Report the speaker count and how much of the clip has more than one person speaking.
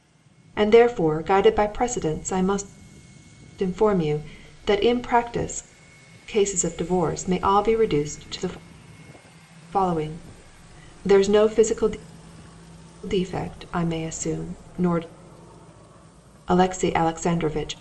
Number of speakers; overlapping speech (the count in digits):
1, no overlap